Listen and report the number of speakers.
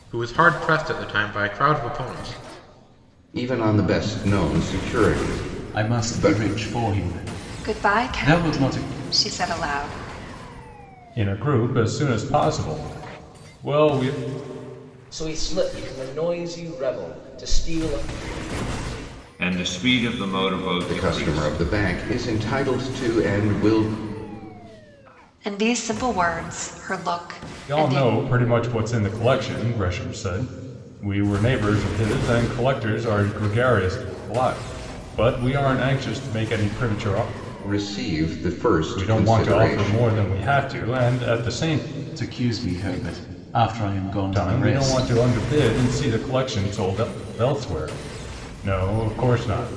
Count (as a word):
seven